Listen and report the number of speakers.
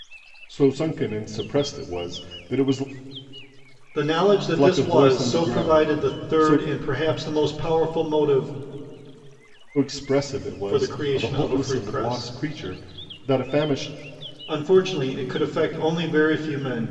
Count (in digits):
2